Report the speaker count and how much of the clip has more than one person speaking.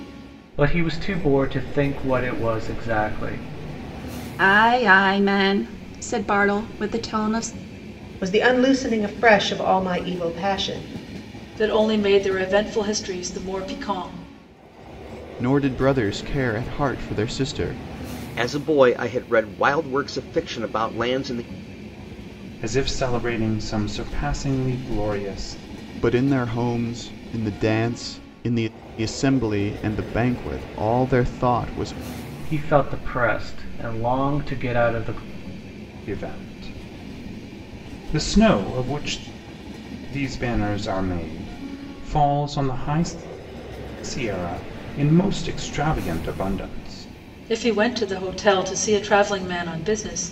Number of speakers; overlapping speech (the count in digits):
7, no overlap